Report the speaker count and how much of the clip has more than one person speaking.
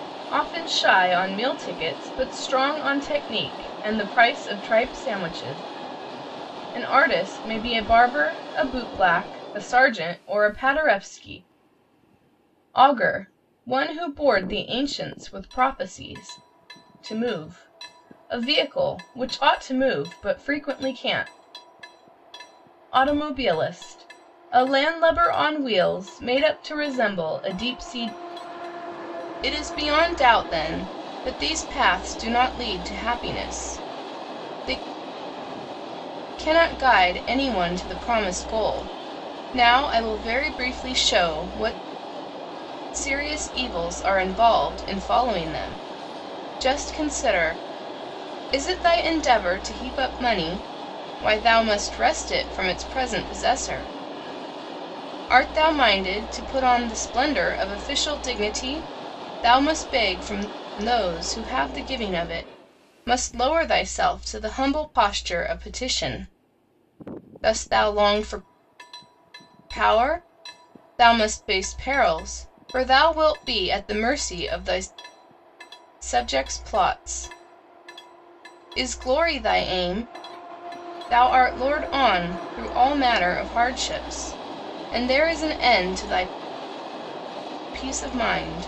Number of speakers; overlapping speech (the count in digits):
1, no overlap